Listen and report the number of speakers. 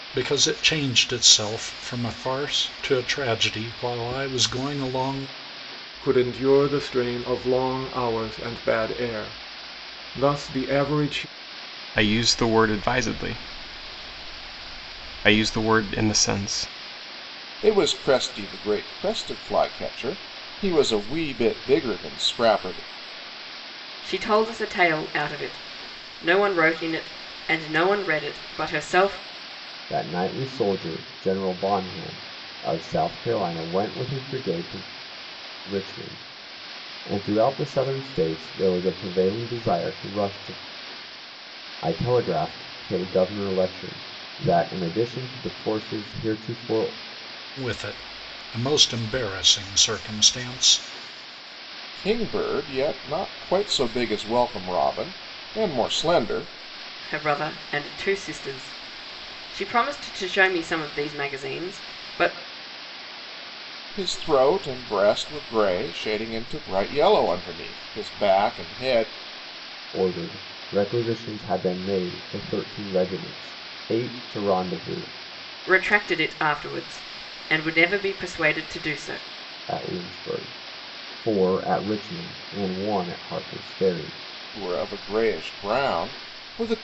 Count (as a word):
six